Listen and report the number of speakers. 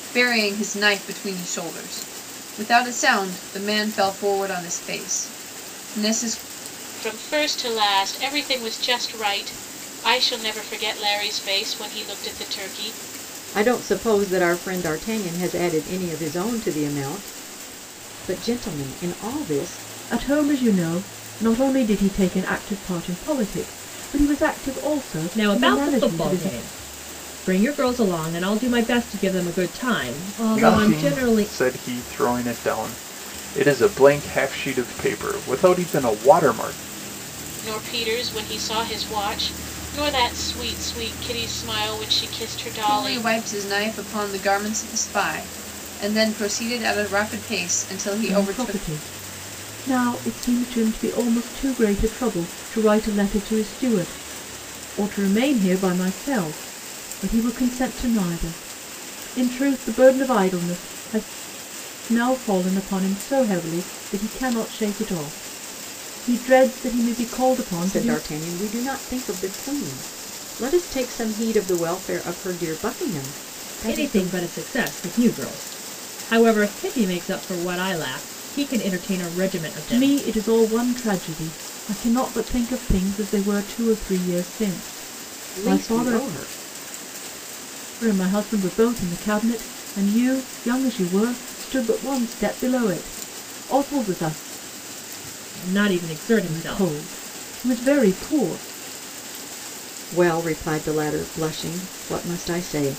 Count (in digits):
6